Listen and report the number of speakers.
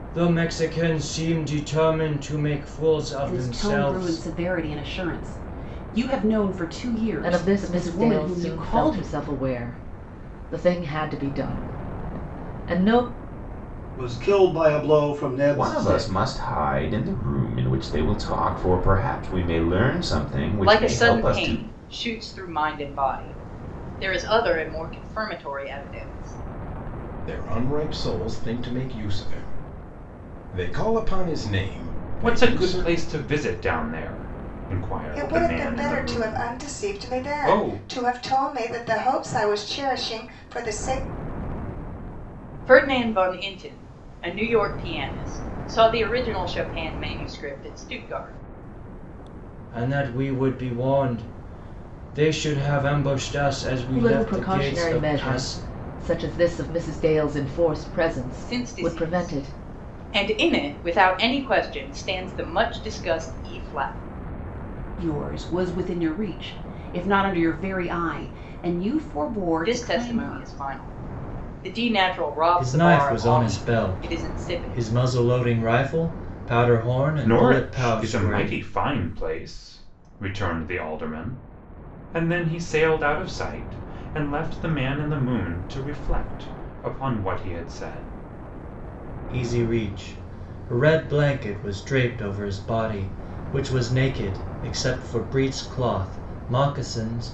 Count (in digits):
9